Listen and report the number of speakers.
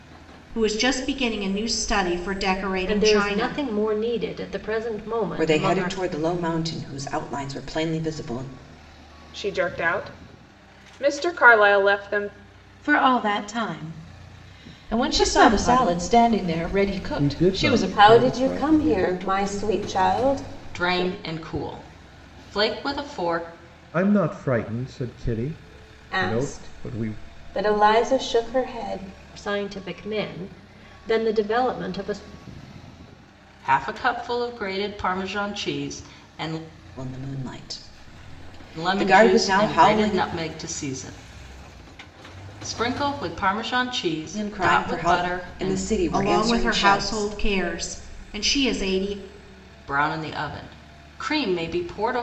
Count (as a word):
nine